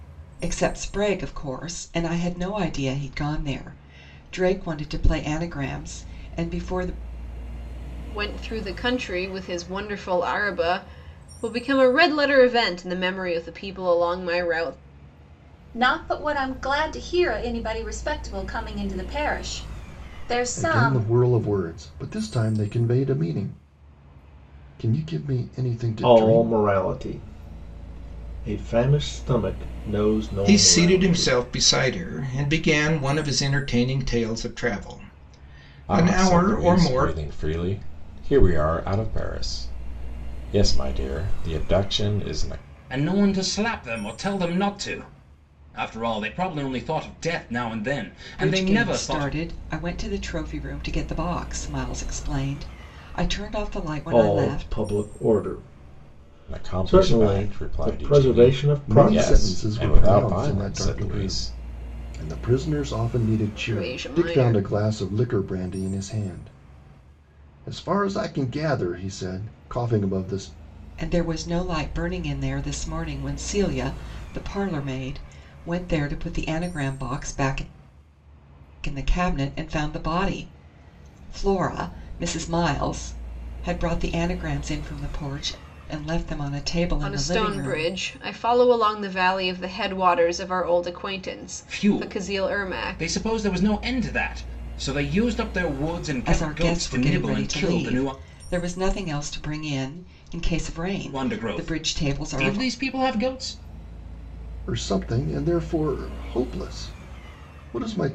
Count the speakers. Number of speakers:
eight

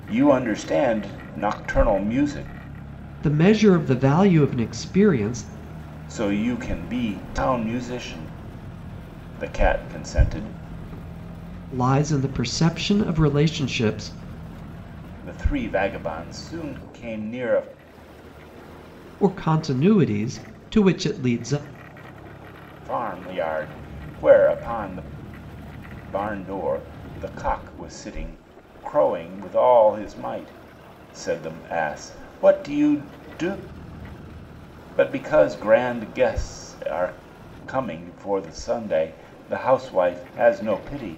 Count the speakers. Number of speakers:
two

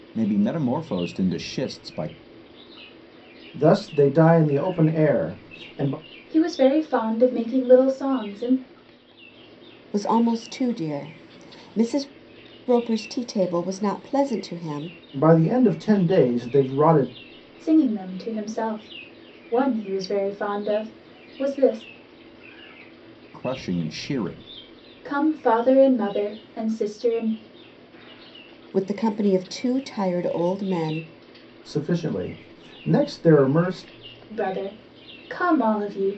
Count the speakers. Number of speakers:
four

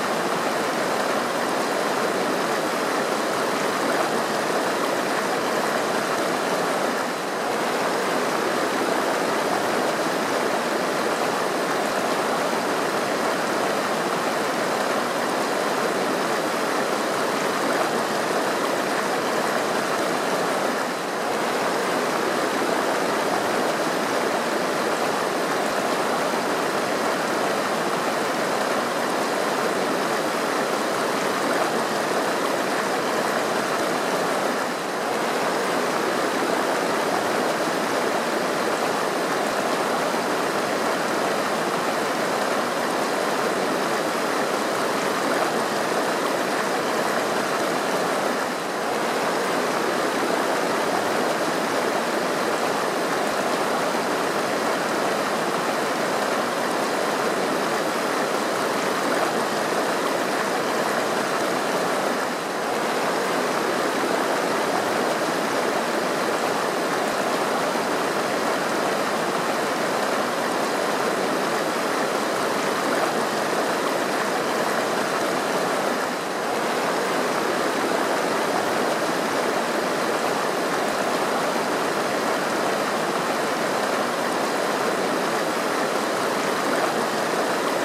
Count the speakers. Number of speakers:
zero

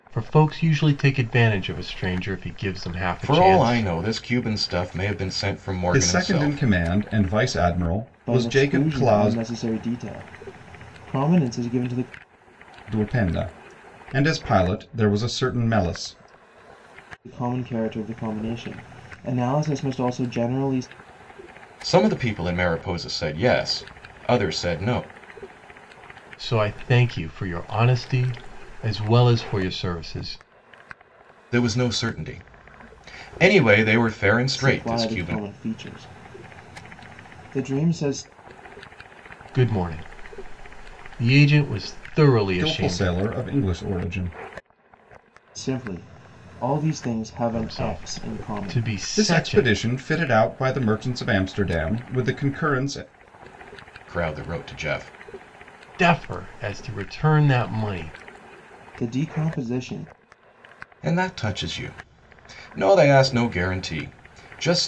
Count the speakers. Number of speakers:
four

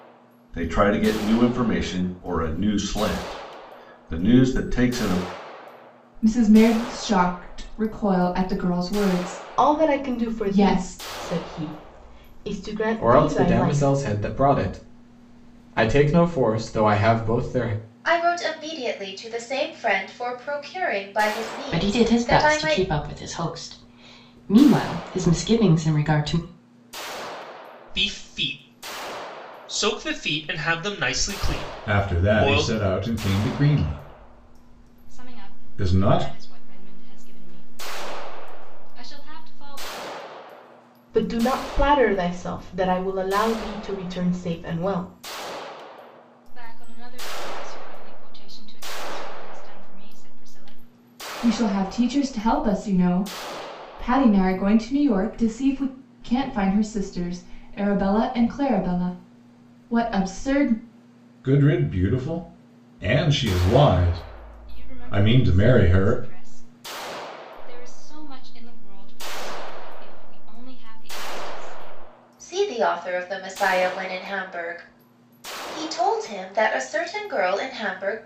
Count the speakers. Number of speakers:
nine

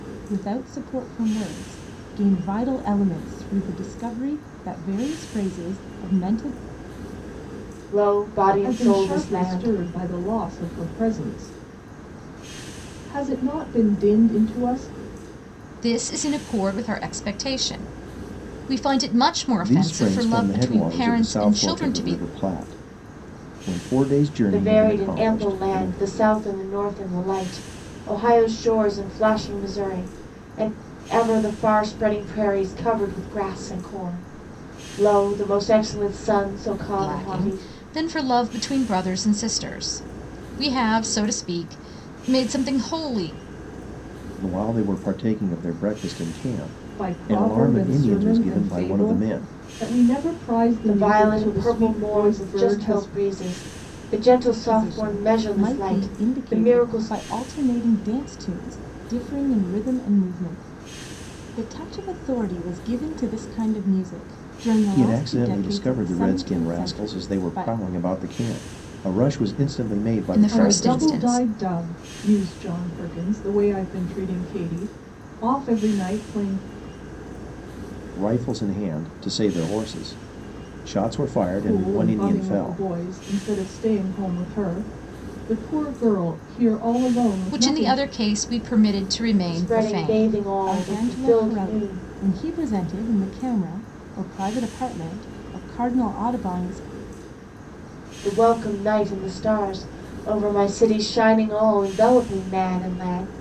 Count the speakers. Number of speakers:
five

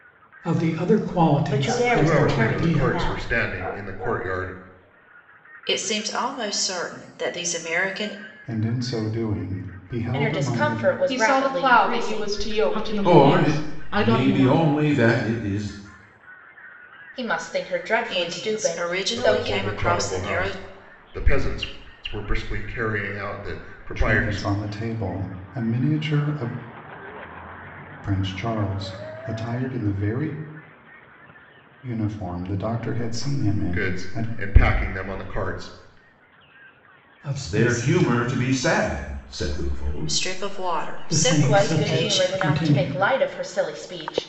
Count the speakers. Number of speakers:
ten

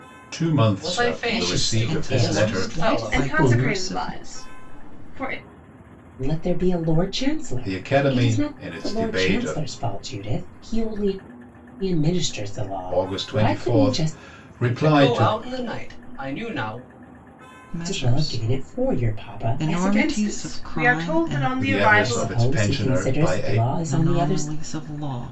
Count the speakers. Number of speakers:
five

